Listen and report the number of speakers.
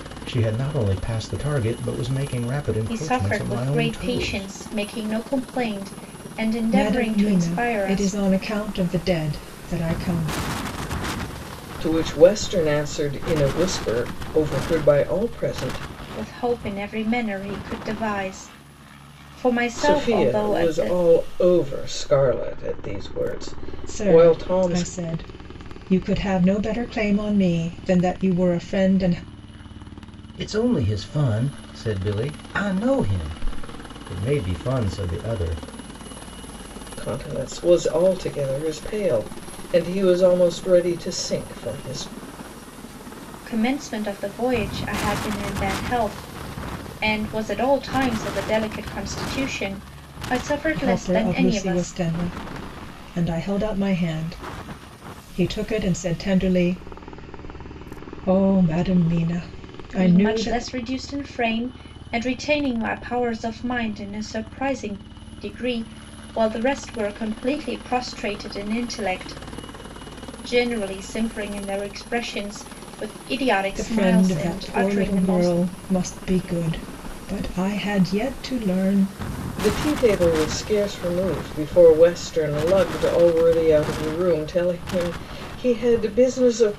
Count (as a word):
four